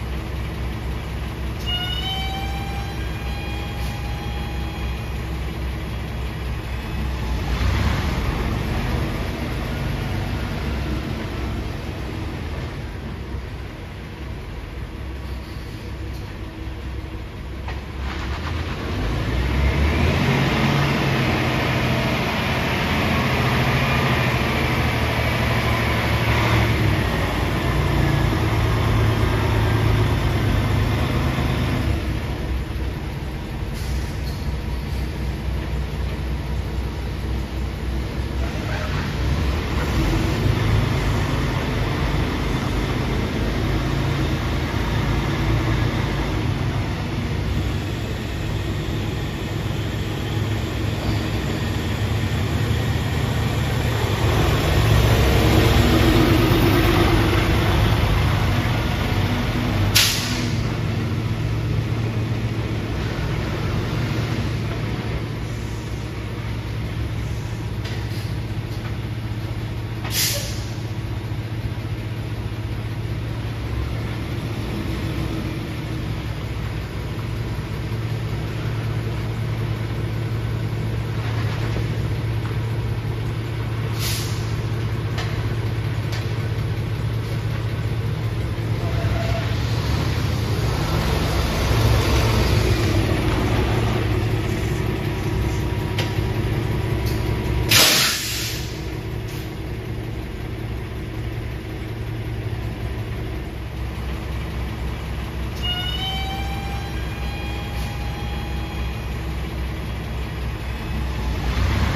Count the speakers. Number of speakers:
0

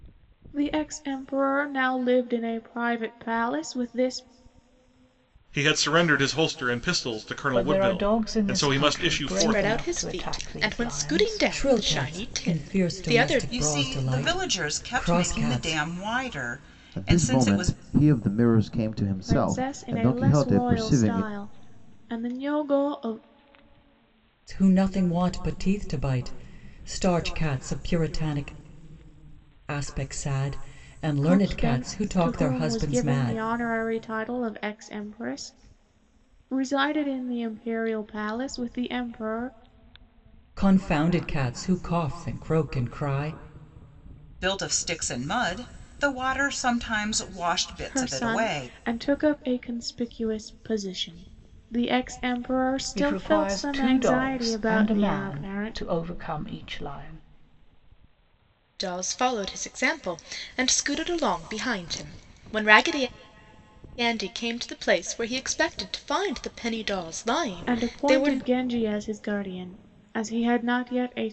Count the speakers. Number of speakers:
7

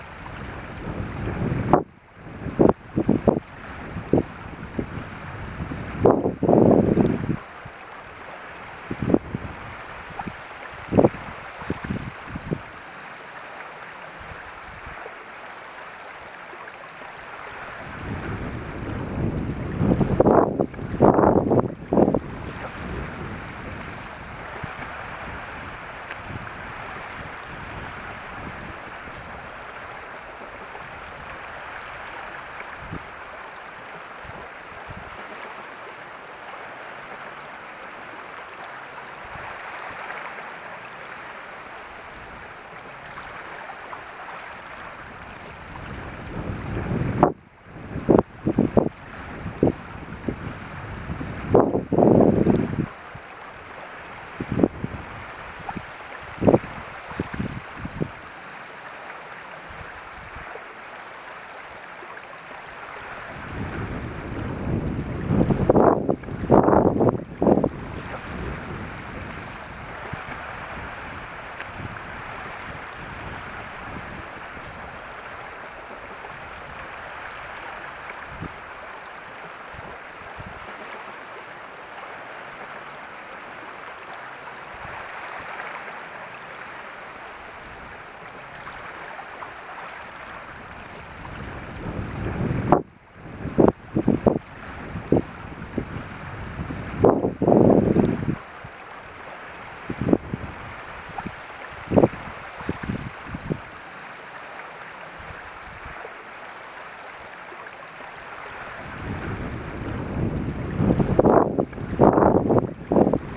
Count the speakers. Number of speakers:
0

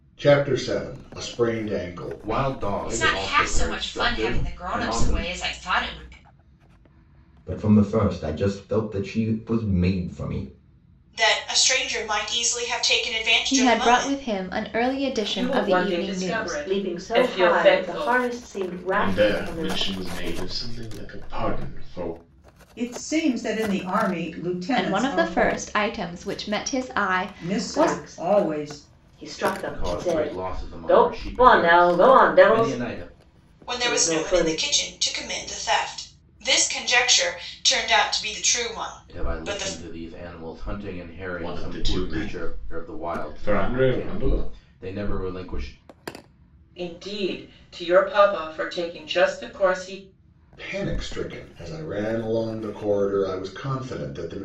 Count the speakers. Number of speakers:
10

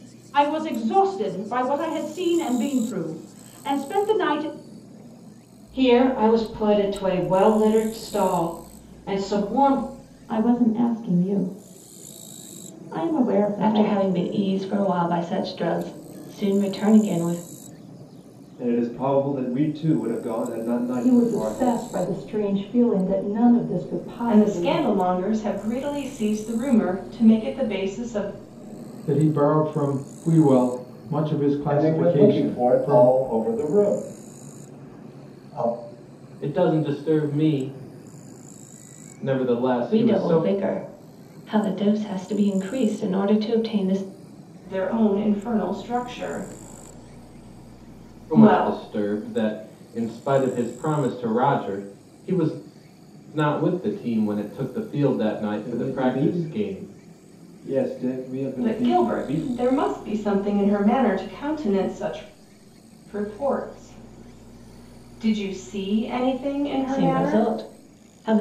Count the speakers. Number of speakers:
10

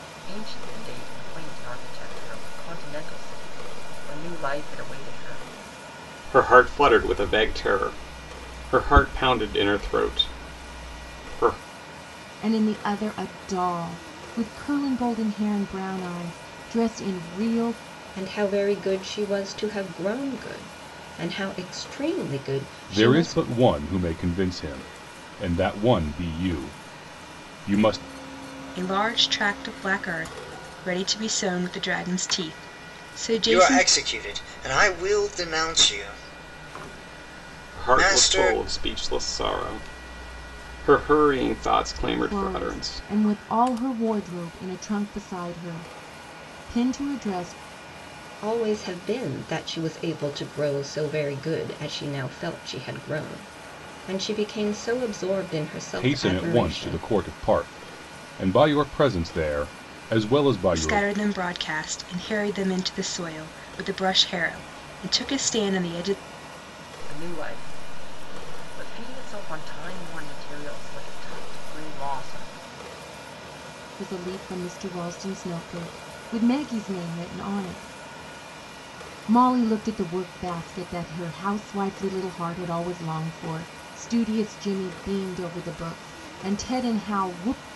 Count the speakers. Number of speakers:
7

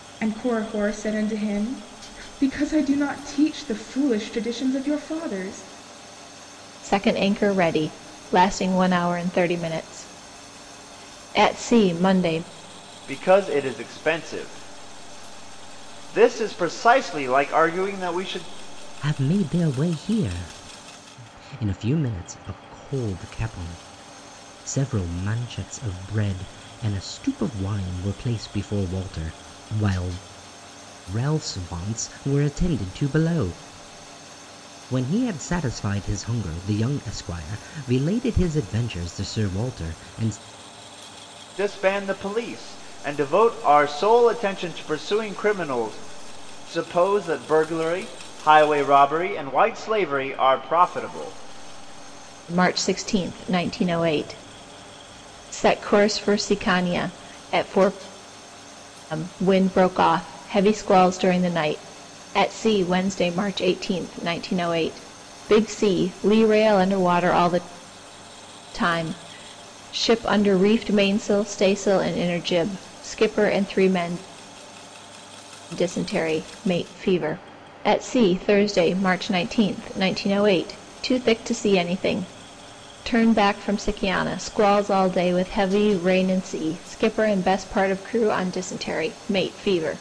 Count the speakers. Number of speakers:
4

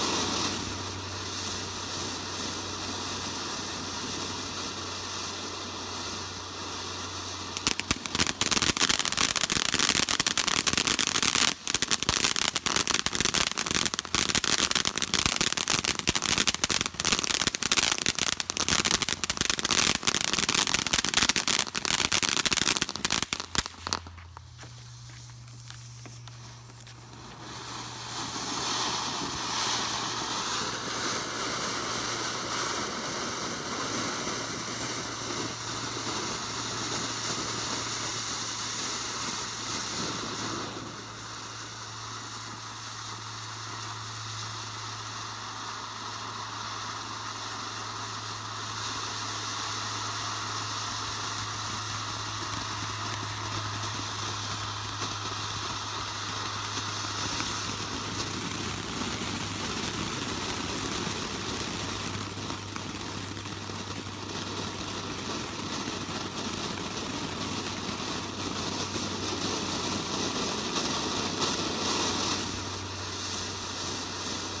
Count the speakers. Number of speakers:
0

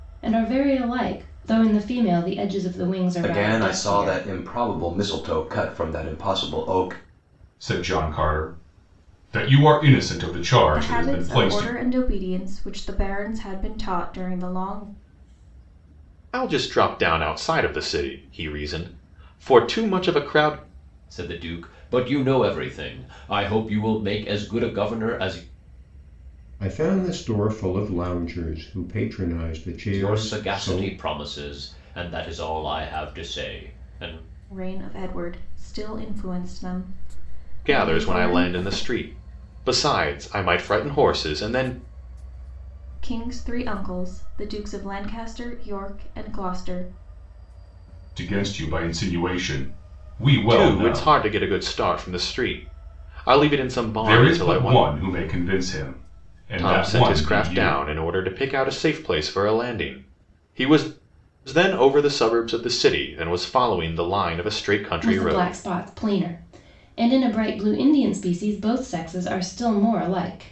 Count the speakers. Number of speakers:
7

